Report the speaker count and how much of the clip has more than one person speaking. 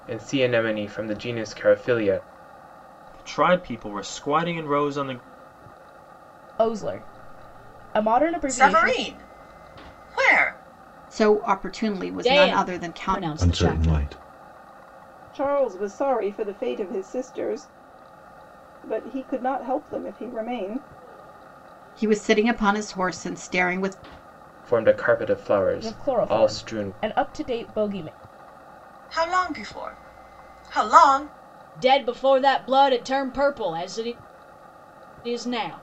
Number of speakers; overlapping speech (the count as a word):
eight, about 10%